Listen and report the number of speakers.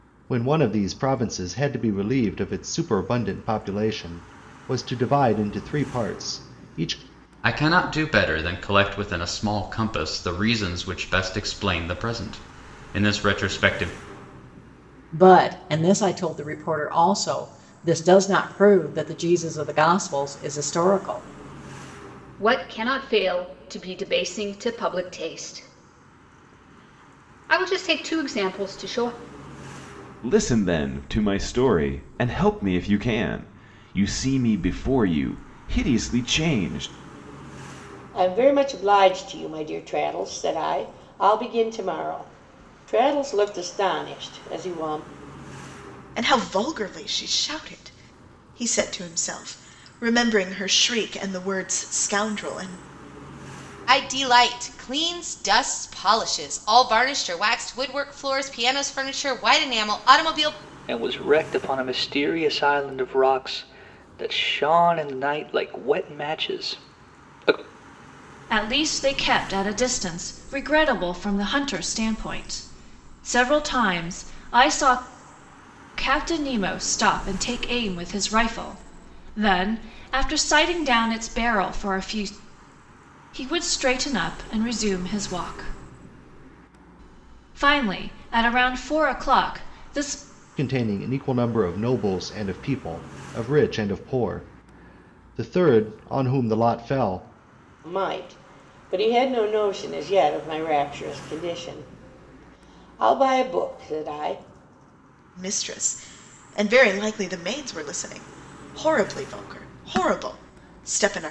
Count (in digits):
10